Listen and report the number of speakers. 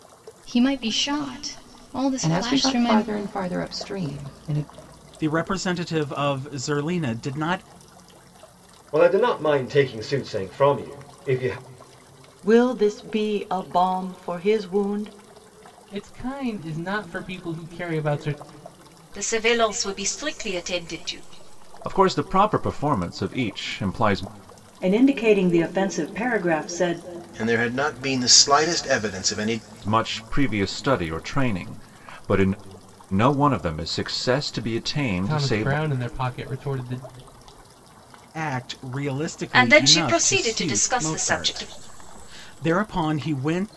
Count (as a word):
ten